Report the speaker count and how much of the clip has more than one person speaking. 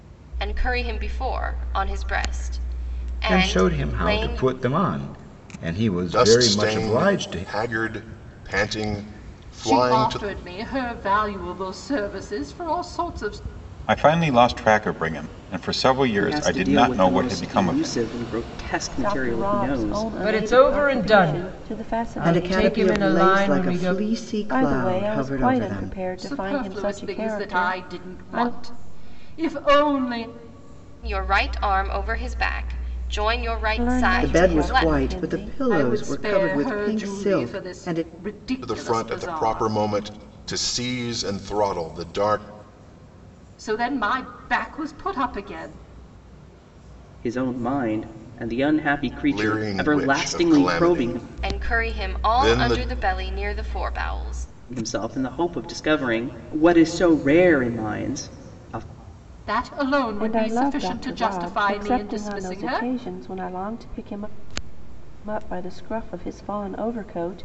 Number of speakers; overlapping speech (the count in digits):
9, about 38%